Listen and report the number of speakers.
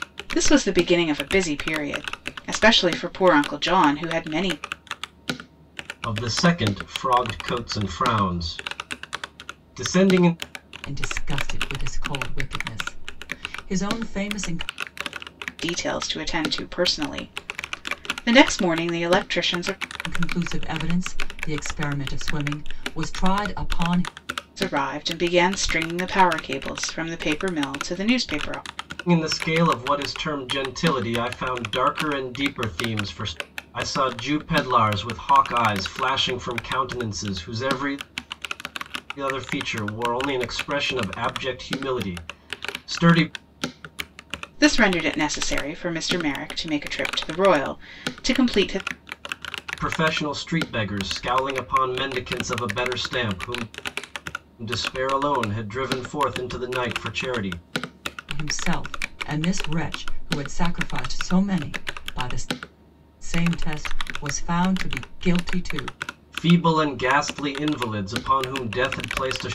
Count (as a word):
three